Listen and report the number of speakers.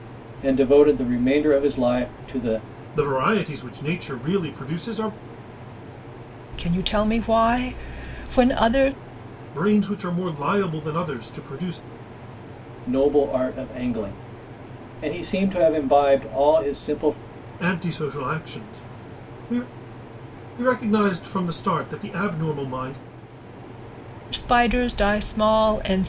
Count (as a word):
three